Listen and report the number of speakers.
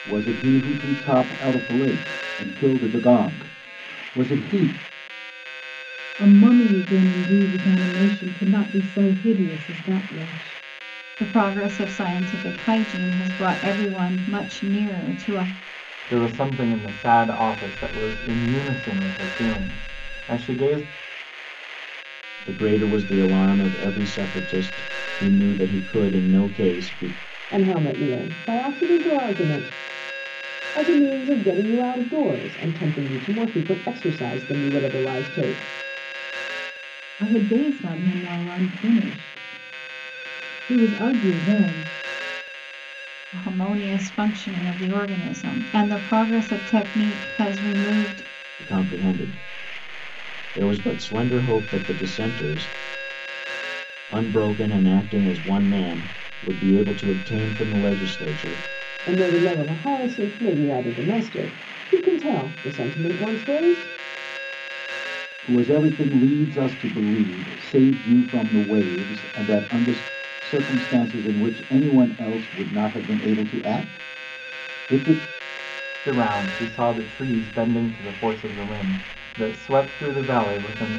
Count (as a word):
six